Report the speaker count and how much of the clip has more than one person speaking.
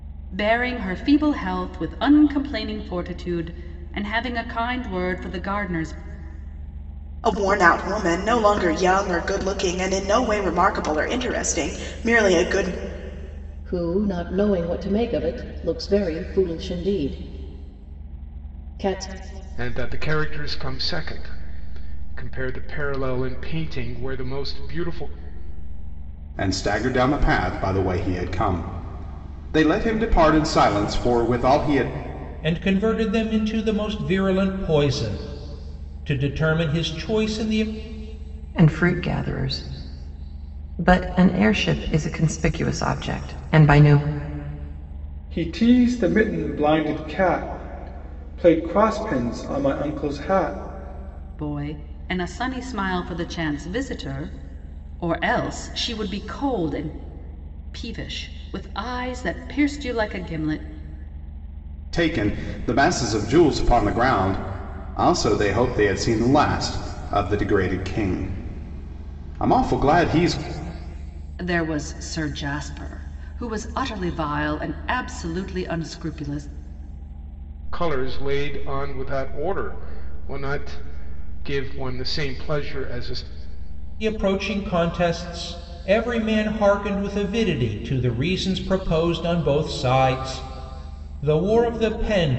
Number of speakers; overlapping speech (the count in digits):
8, no overlap